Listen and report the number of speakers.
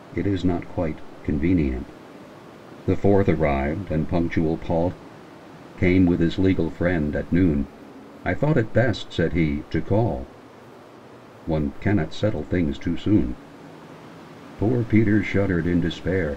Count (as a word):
one